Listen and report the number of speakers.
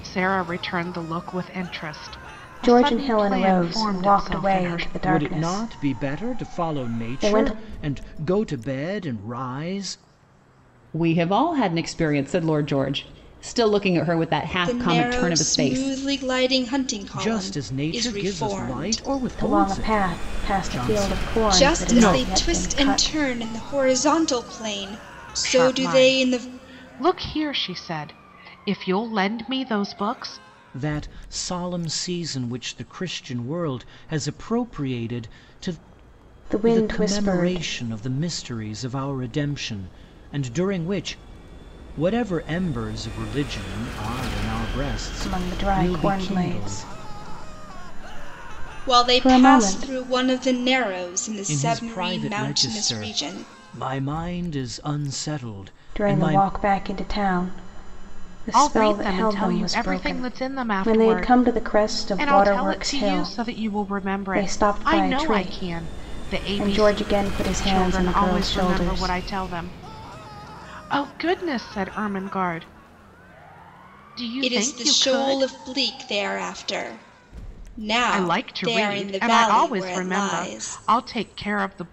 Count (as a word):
five